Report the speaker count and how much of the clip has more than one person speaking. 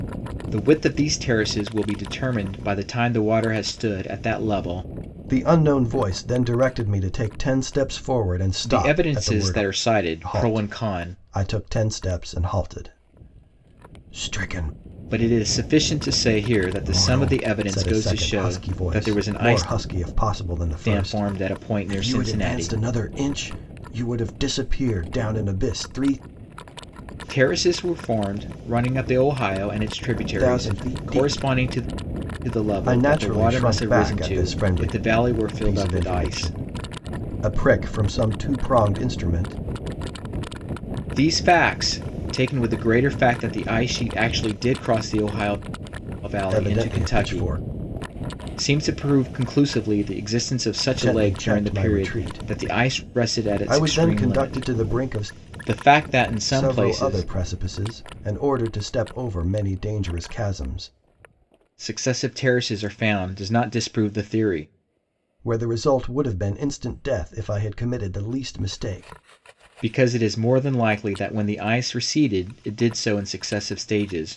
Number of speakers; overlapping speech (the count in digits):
2, about 23%